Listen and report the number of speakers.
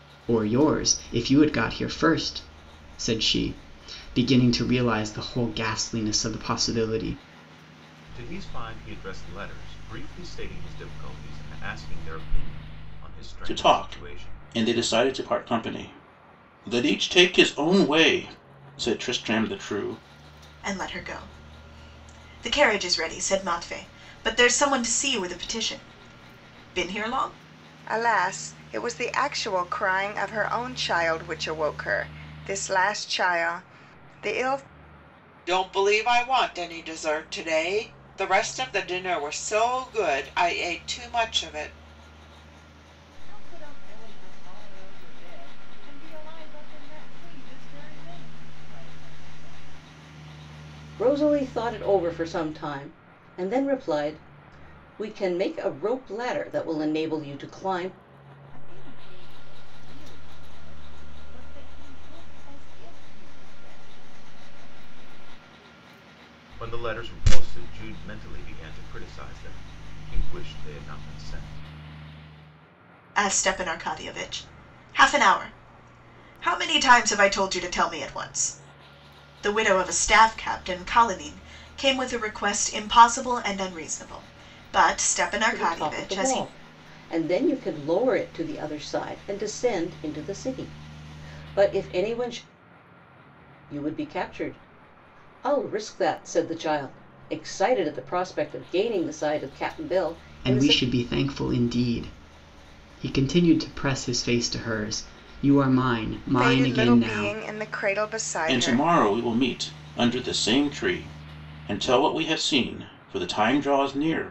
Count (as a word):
eight